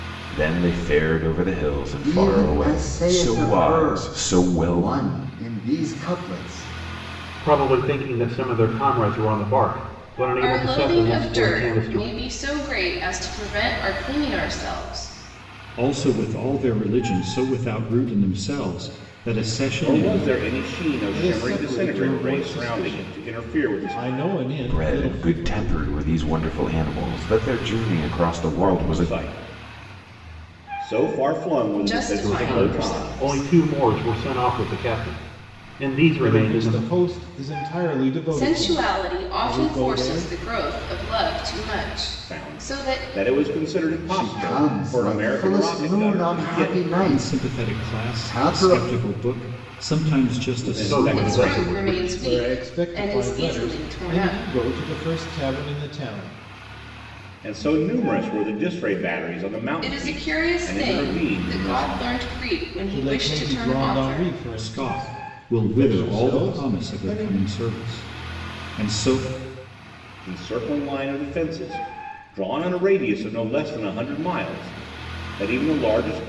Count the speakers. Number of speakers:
seven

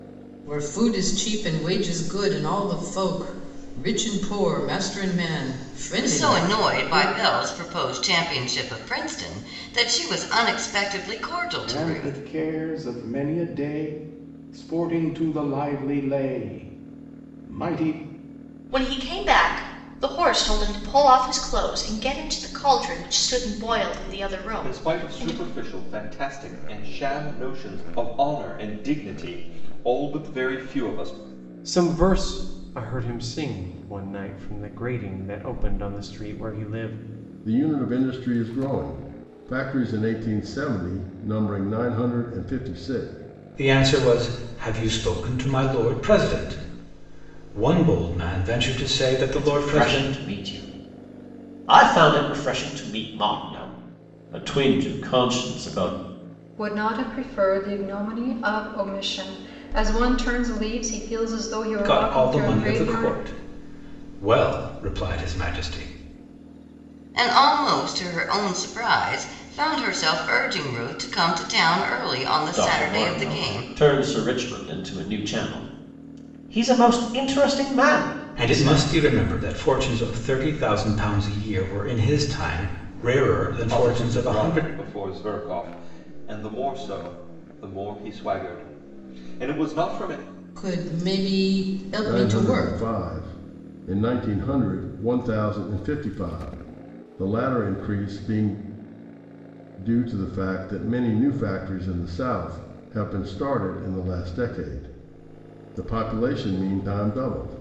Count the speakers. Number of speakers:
ten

